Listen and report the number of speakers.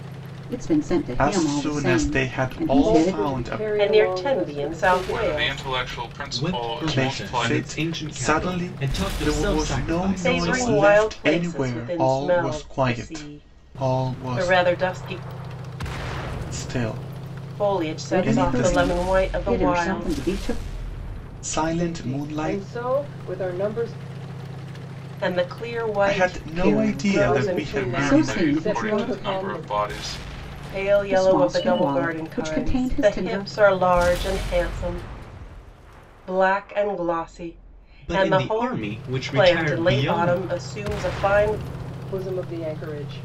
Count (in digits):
6